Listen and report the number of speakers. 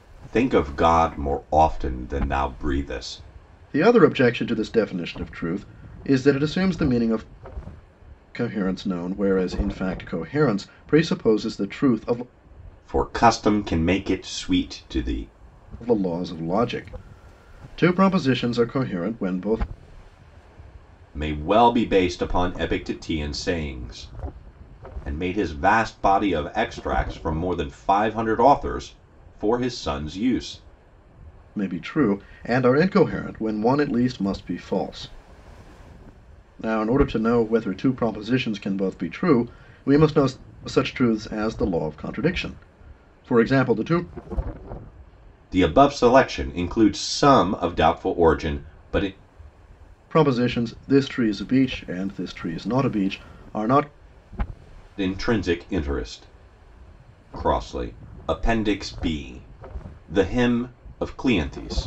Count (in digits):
2